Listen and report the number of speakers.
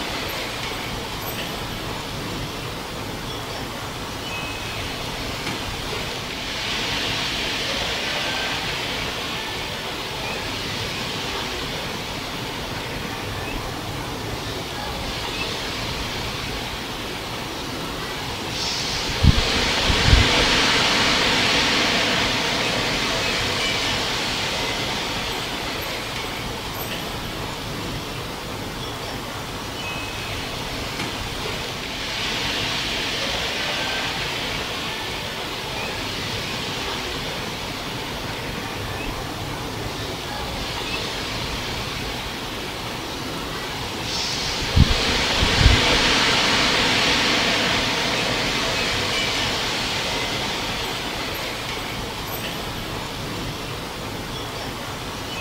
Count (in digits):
0